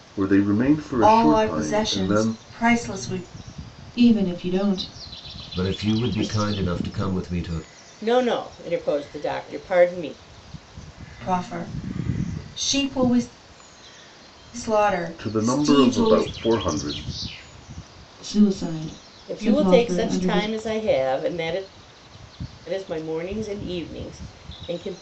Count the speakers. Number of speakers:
5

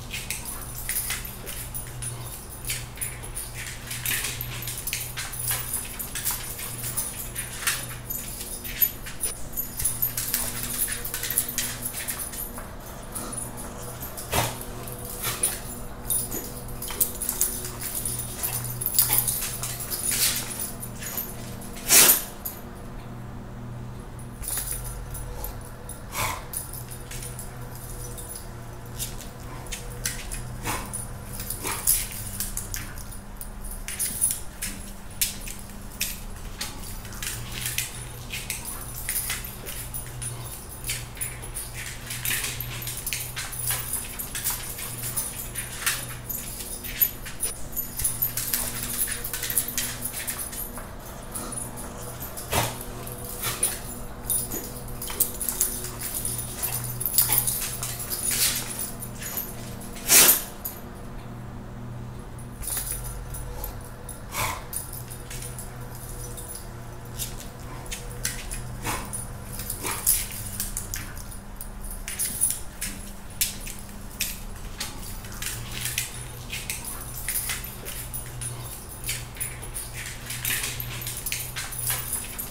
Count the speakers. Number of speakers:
0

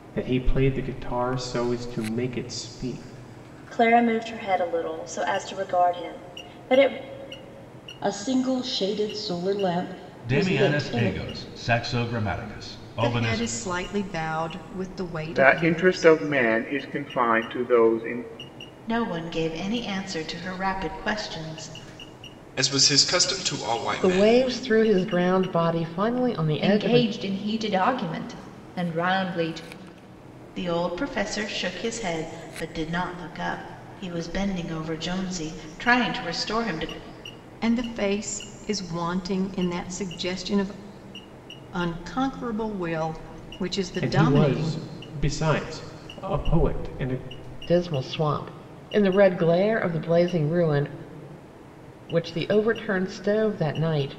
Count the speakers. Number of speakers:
10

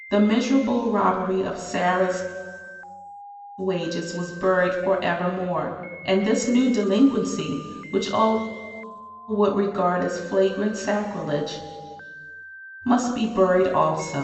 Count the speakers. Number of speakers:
1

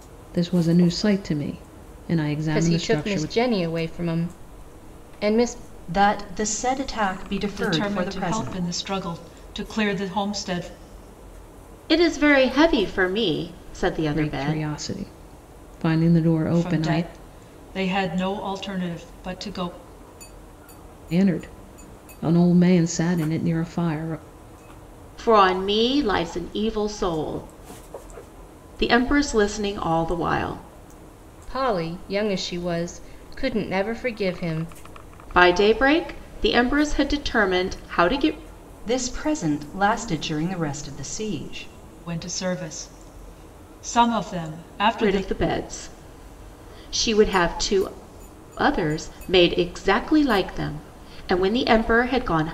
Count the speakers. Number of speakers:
5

